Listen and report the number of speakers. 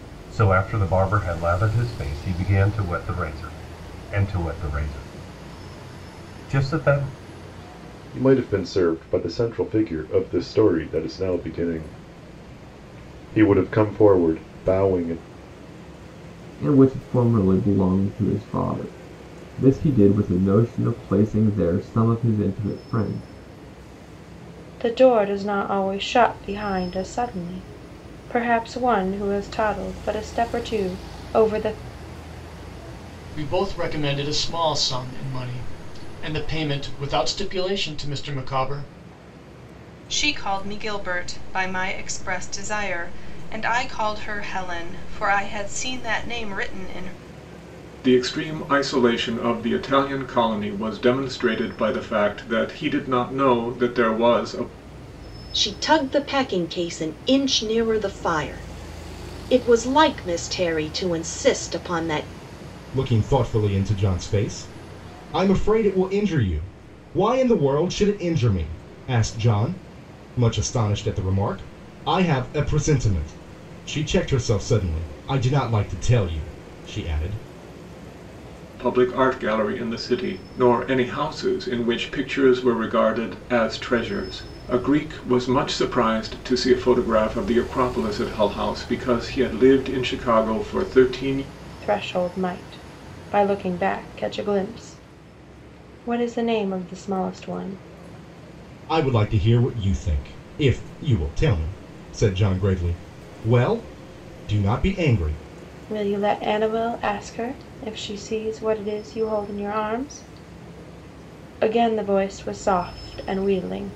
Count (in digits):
9